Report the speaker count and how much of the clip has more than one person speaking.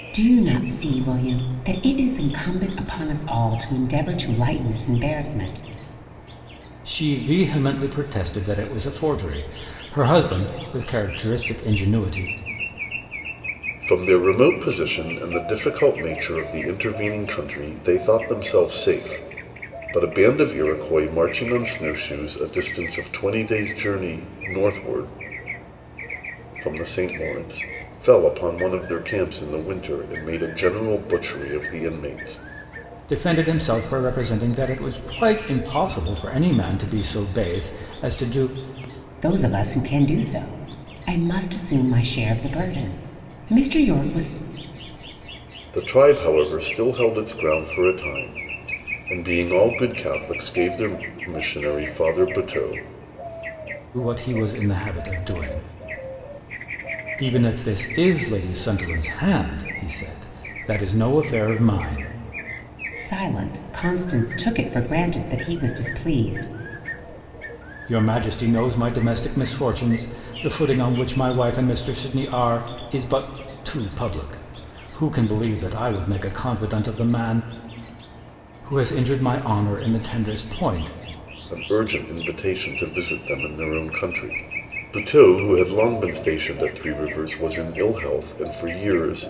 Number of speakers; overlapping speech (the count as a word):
three, no overlap